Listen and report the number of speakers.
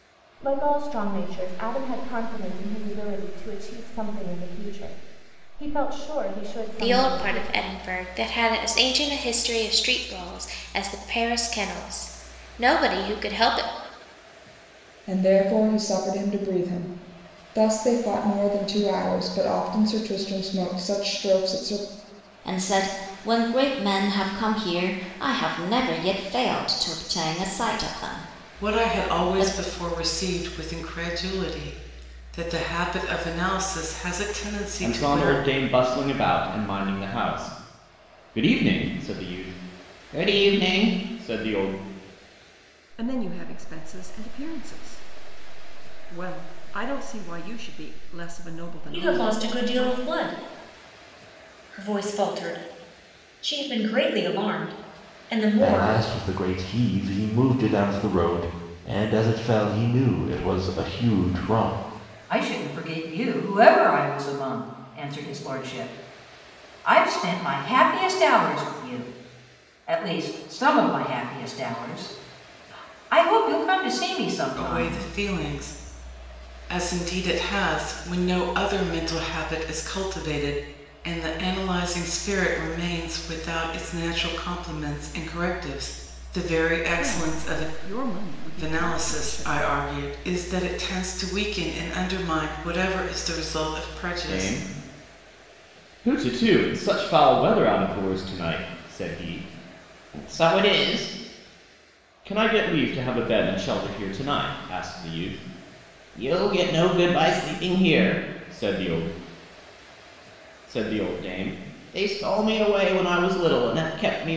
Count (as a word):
ten